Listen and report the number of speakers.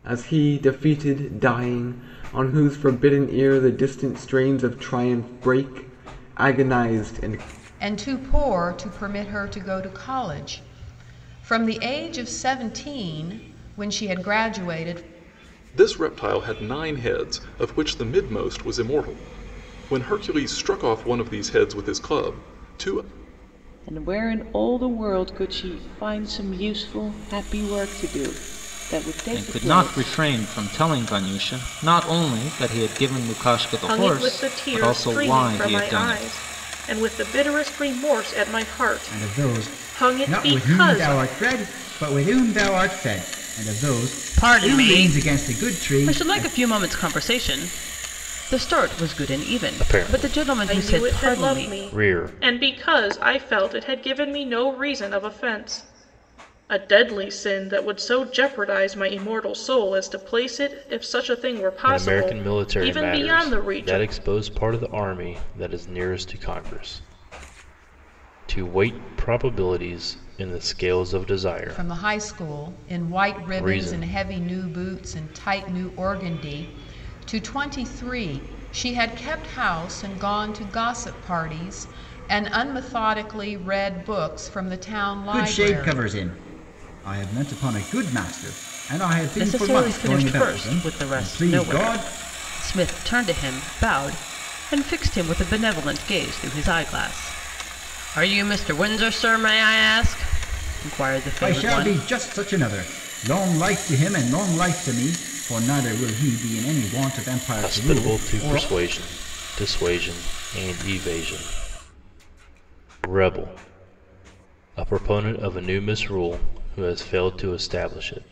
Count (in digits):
9